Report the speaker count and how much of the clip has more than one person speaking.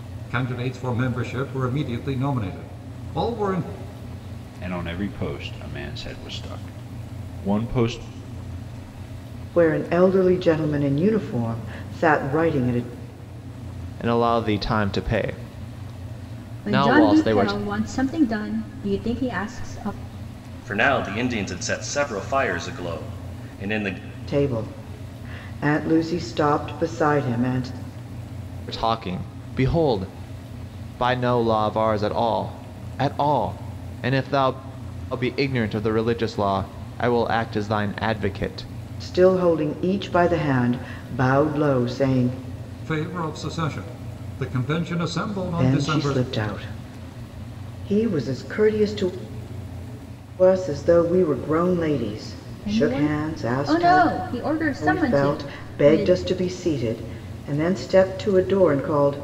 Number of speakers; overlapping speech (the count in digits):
6, about 8%